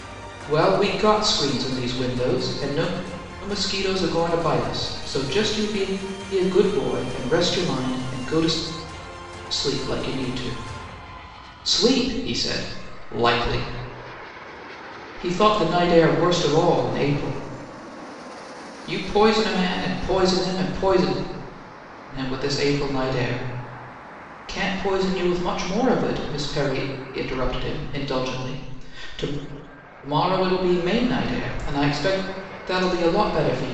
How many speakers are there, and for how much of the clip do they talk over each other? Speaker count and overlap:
one, no overlap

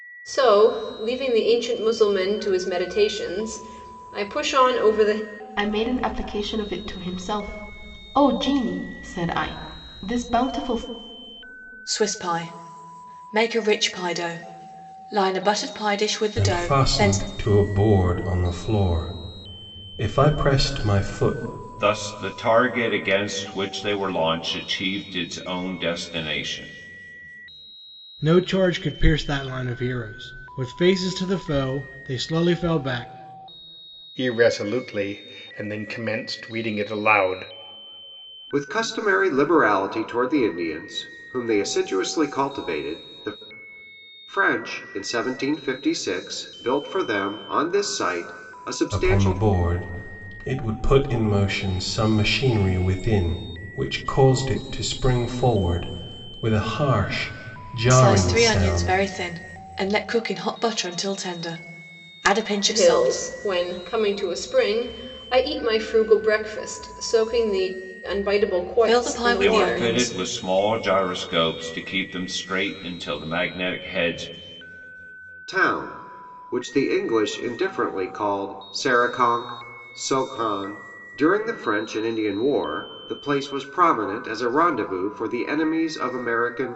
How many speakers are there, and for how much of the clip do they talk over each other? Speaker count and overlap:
eight, about 5%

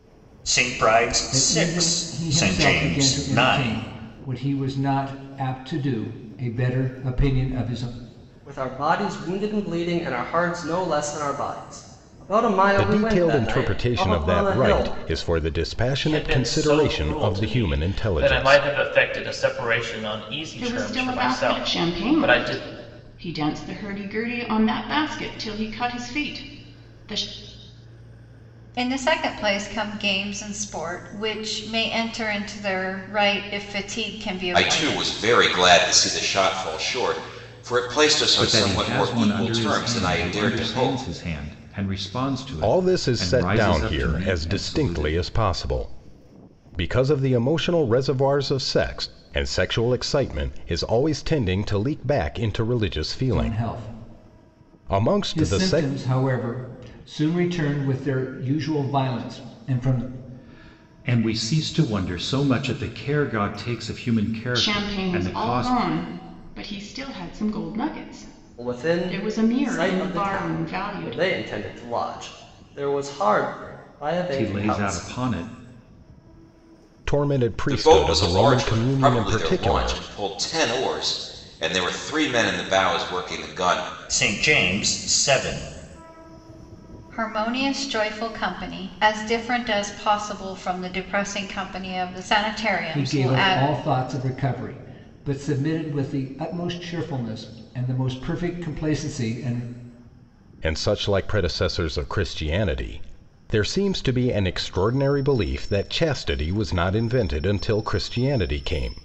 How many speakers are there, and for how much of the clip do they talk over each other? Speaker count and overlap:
nine, about 25%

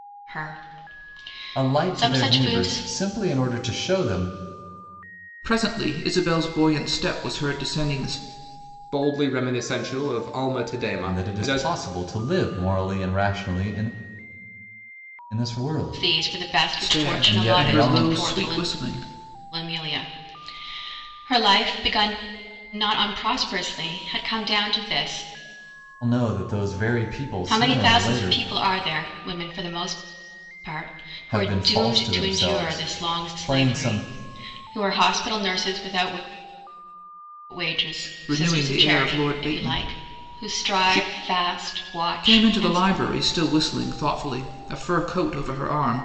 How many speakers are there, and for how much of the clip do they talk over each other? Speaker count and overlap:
four, about 26%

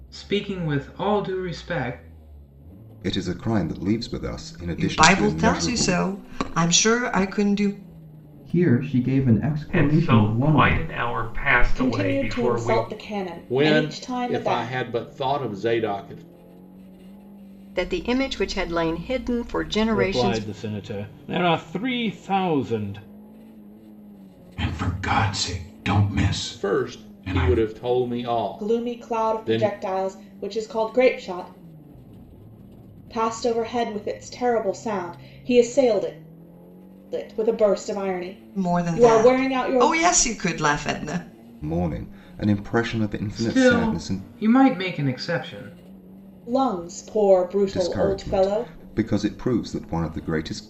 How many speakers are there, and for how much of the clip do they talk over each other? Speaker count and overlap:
ten, about 22%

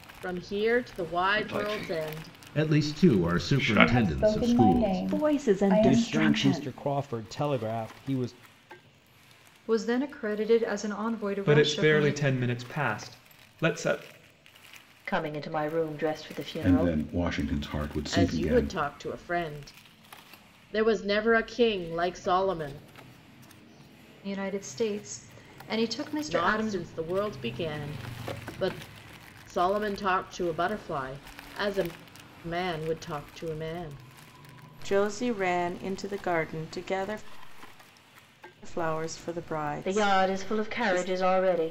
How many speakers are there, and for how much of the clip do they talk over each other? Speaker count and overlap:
ten, about 21%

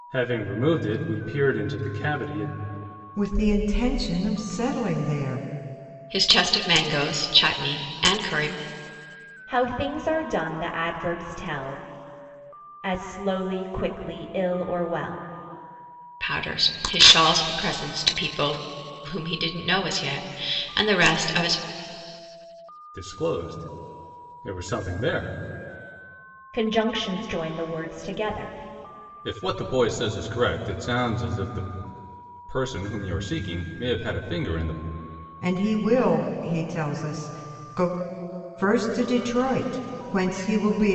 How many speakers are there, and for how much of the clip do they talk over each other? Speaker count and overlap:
four, no overlap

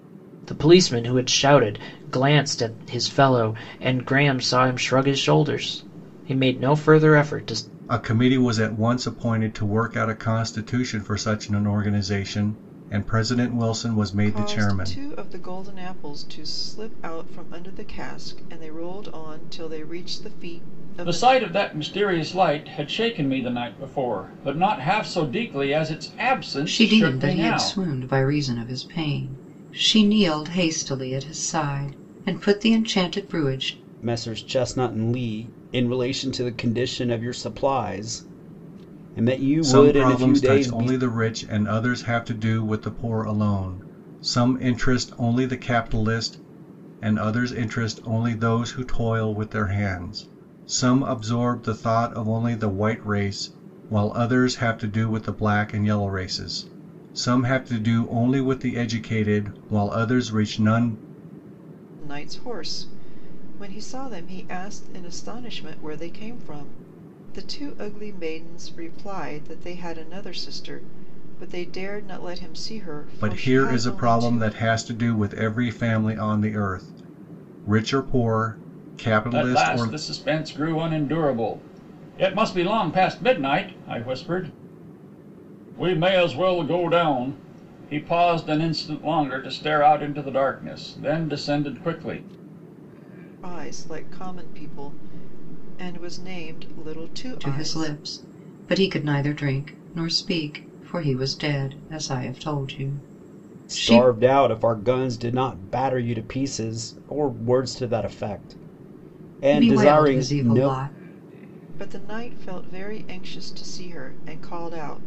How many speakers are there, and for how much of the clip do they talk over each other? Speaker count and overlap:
six, about 7%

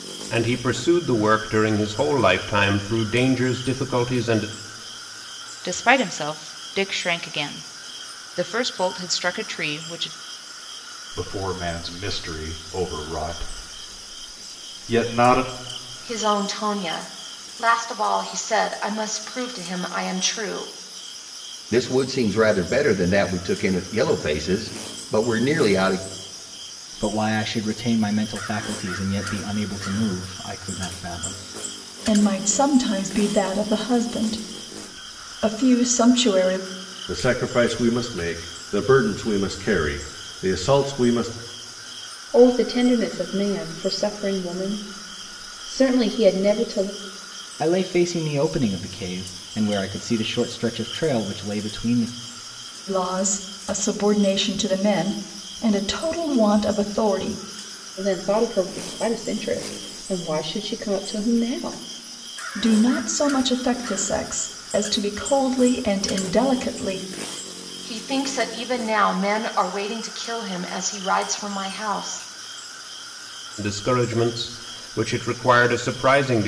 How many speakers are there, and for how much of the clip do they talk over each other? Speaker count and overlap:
nine, no overlap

